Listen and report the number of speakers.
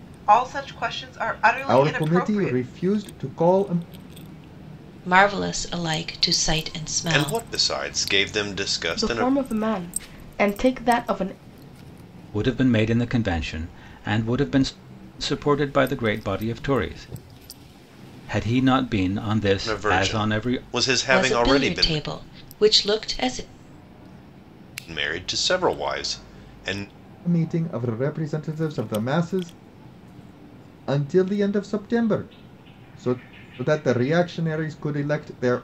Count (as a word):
six